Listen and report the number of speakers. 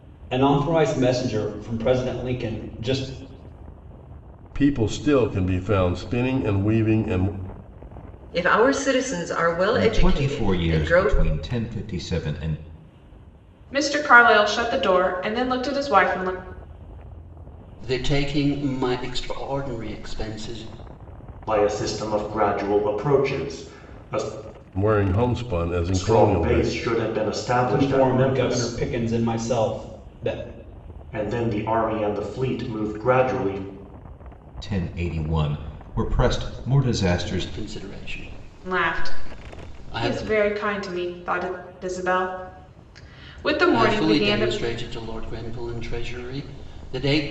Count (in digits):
7